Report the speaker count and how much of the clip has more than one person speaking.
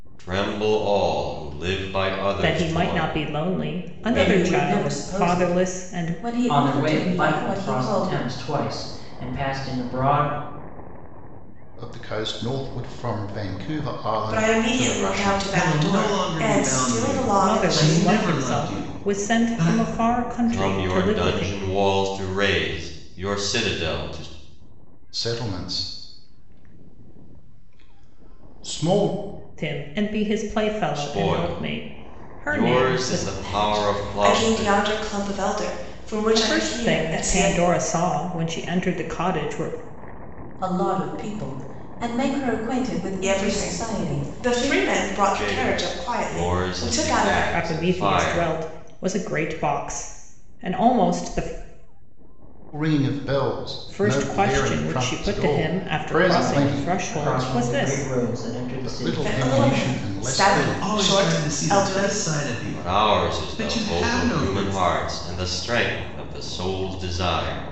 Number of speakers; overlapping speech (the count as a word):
seven, about 47%